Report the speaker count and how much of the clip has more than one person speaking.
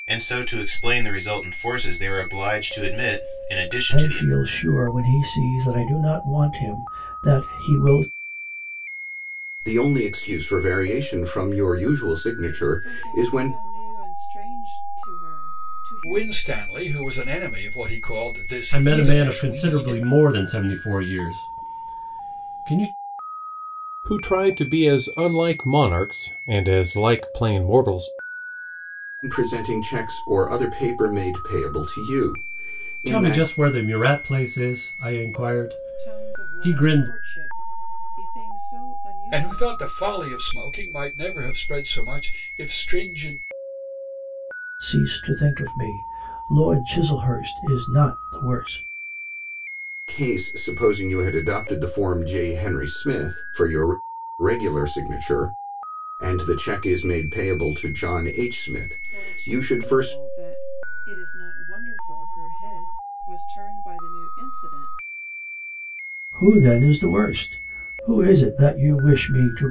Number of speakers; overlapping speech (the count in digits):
7, about 10%